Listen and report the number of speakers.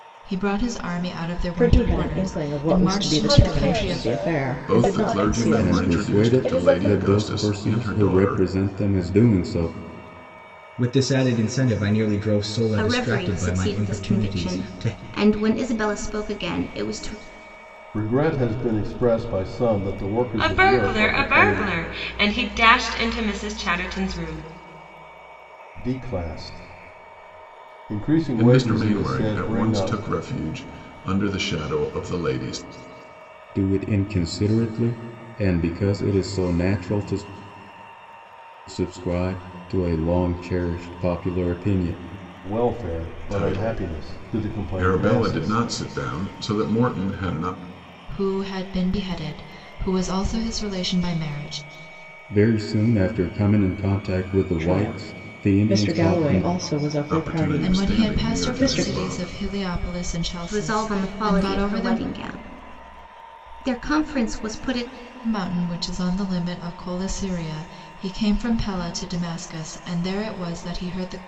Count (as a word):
nine